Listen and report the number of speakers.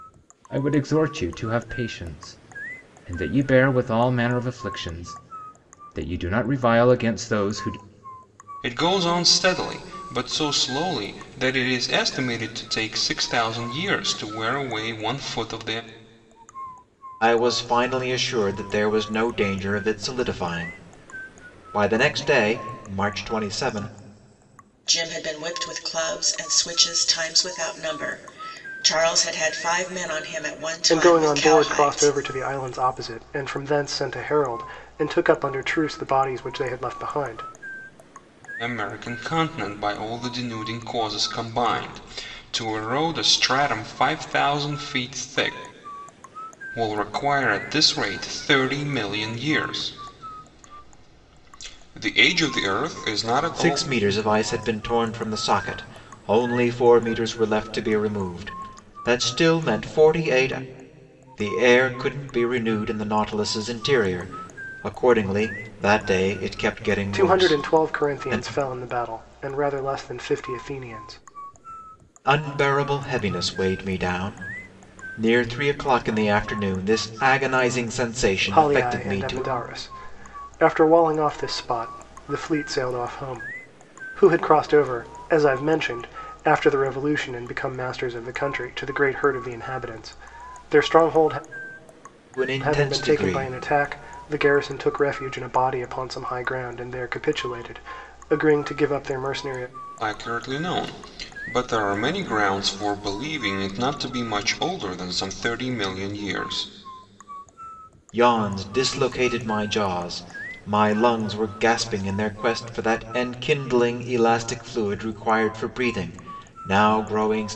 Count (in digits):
5